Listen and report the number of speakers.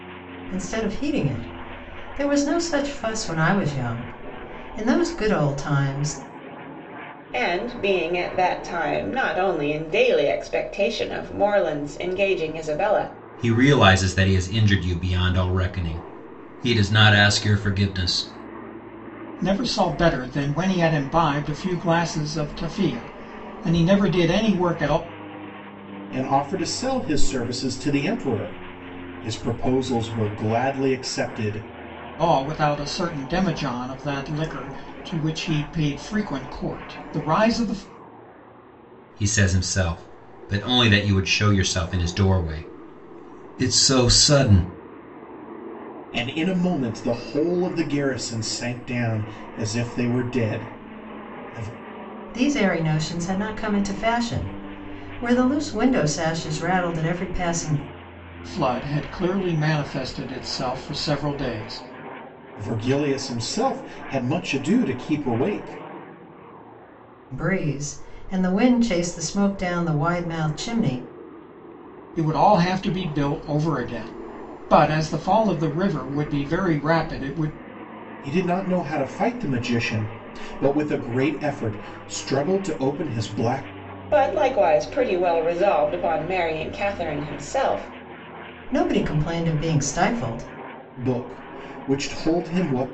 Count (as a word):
five